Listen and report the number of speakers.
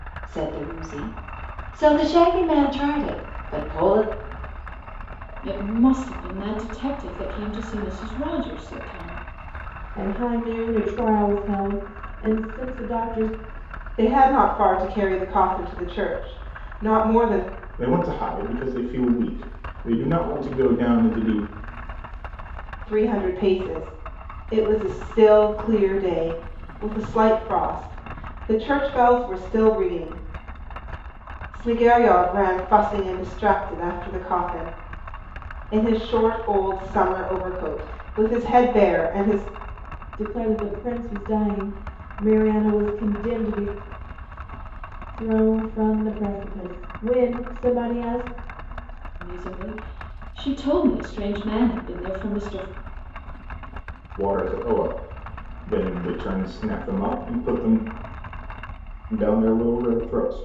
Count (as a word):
five